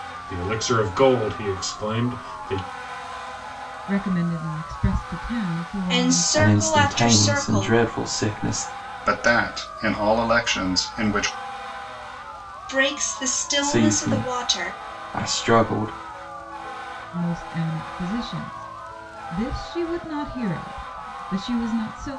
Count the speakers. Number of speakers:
five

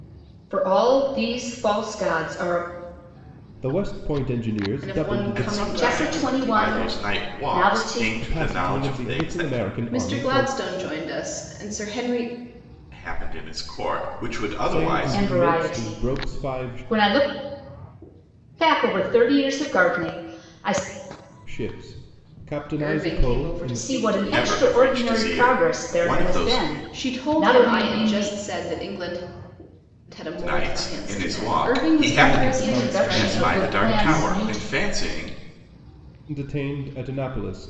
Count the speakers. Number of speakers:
four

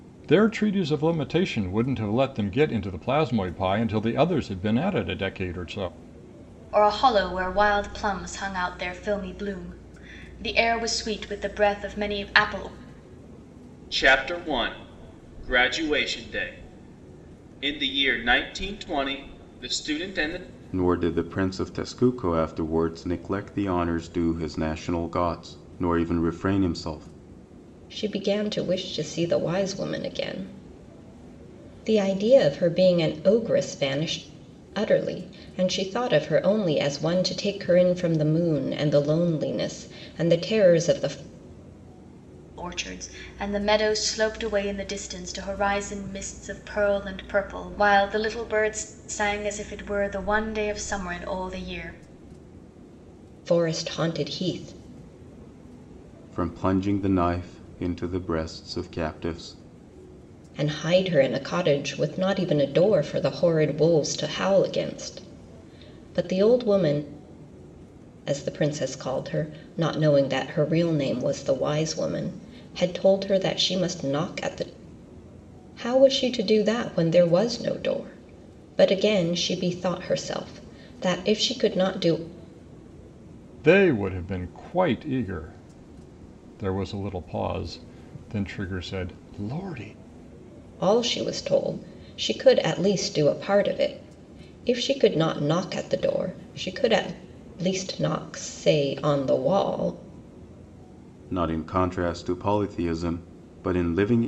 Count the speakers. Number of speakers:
five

